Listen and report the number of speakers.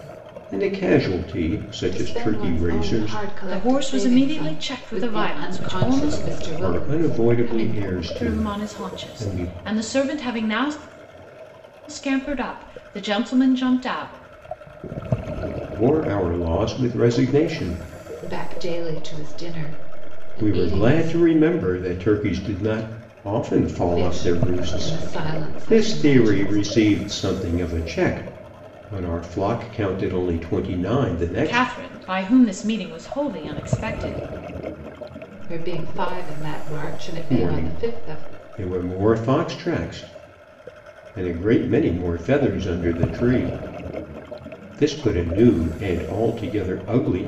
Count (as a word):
three